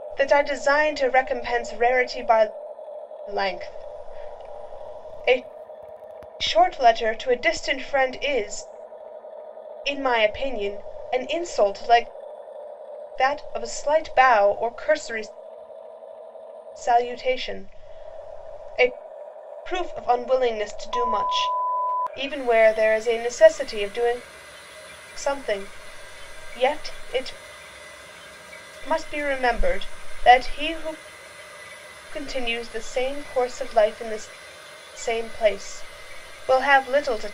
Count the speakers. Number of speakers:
one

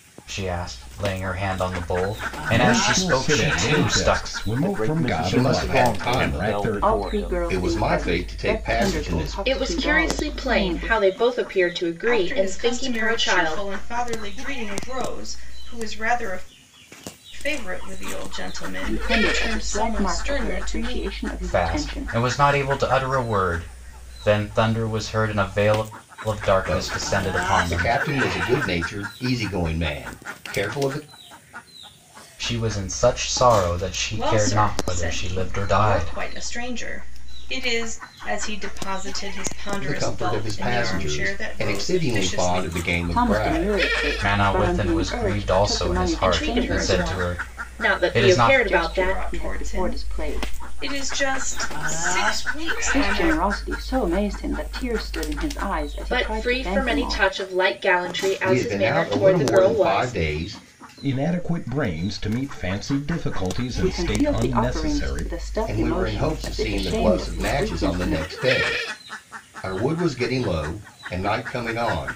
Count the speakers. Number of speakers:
seven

